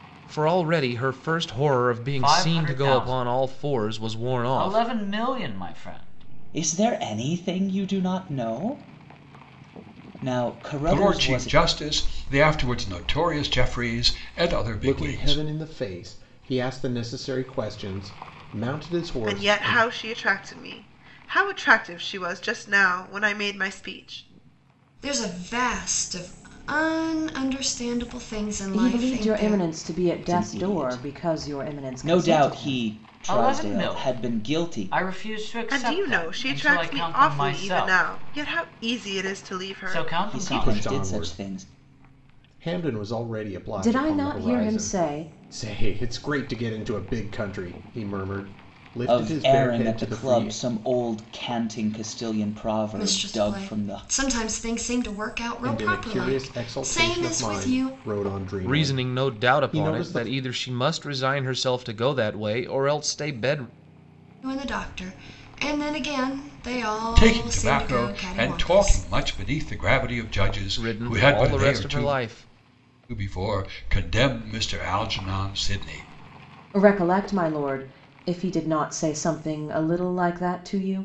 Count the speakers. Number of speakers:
8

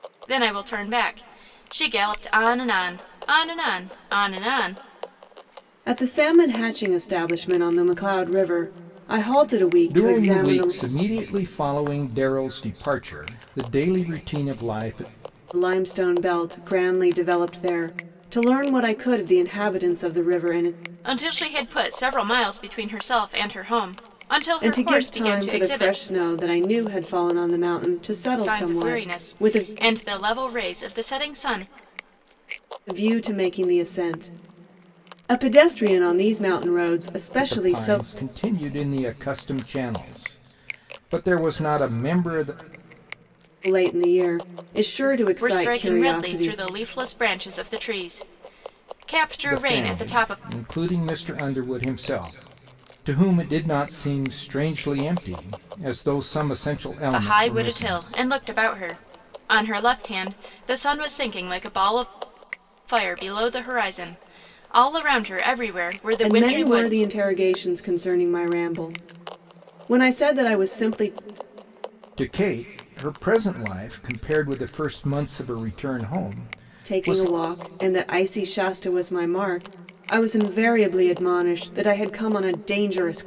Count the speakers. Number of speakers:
3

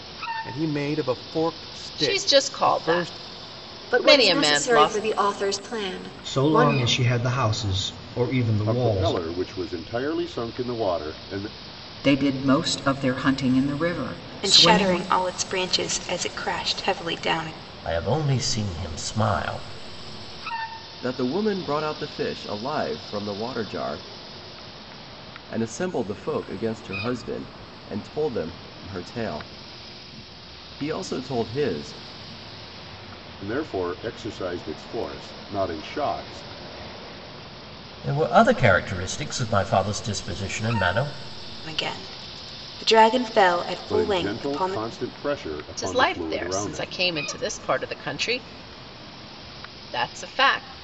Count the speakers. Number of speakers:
9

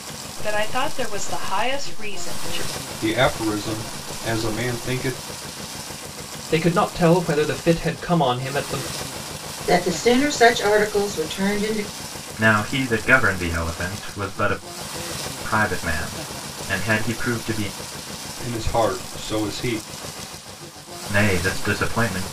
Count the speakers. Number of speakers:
5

